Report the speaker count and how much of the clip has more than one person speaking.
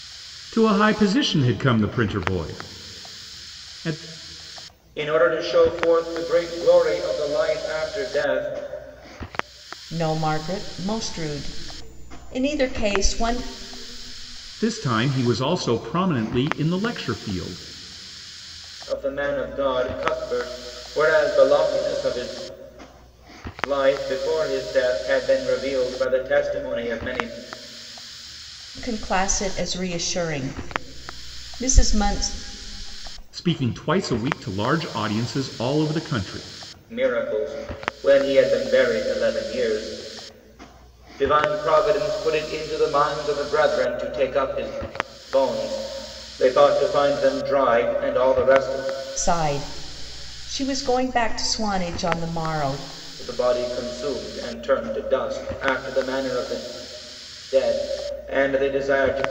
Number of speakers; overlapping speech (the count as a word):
three, no overlap